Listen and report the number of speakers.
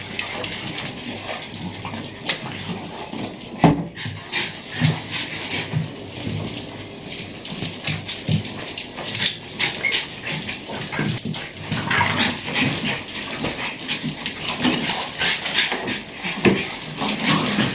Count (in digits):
0